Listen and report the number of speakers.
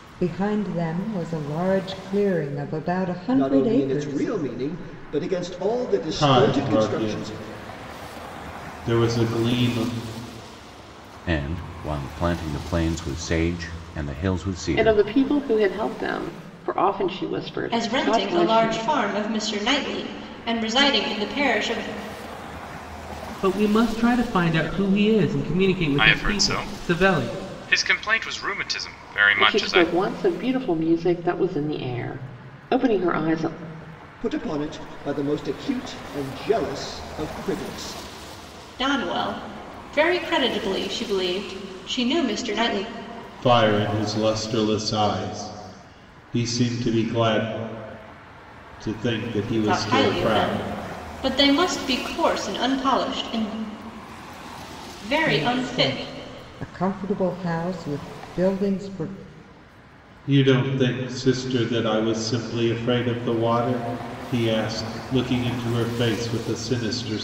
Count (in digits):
8